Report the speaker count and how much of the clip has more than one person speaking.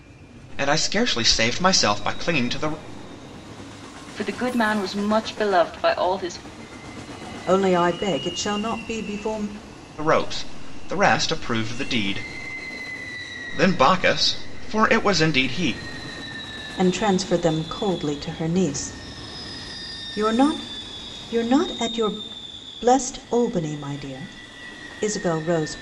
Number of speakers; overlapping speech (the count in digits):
3, no overlap